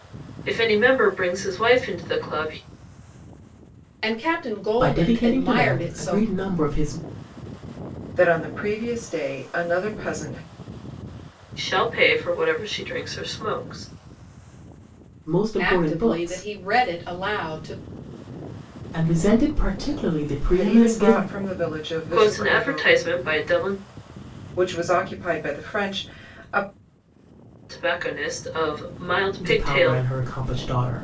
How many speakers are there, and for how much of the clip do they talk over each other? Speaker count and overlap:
4, about 15%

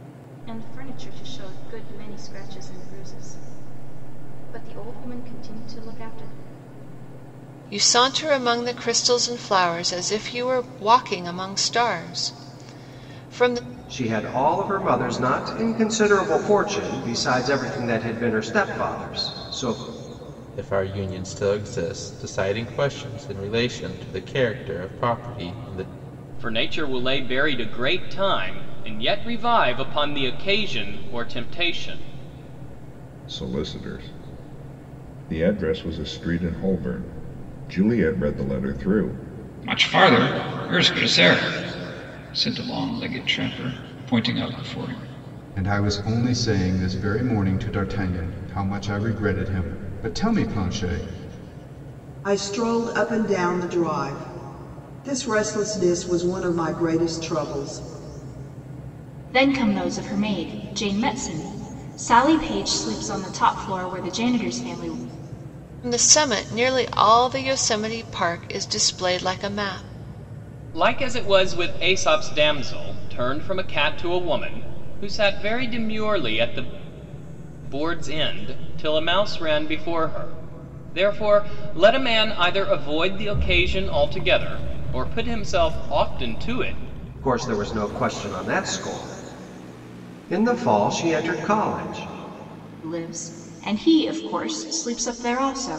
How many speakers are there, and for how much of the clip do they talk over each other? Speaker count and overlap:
10, no overlap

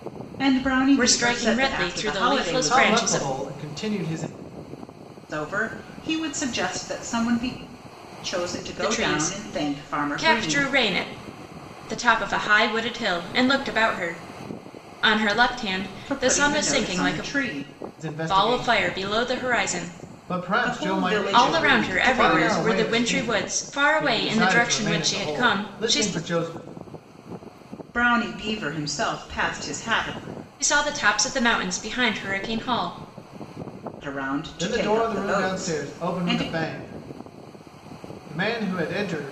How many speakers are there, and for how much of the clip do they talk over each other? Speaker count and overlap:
3, about 35%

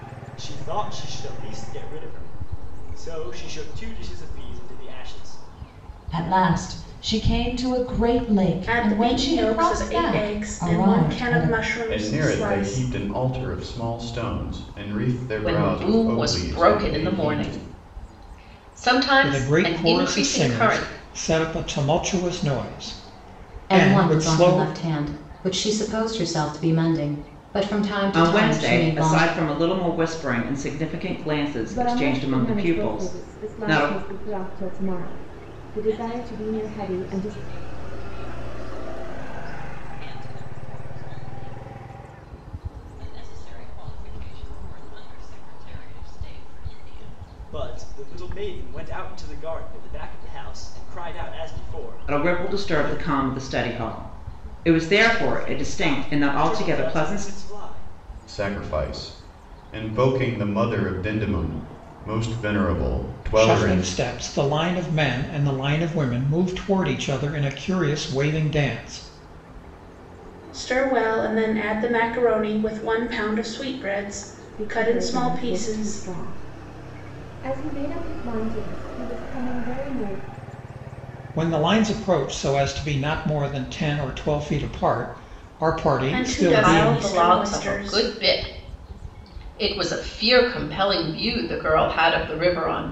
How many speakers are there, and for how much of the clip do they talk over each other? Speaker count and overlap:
10, about 23%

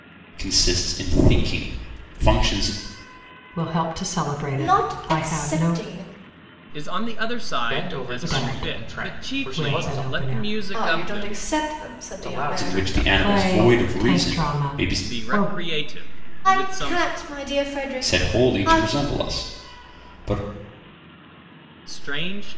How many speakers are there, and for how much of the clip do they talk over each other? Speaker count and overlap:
5, about 42%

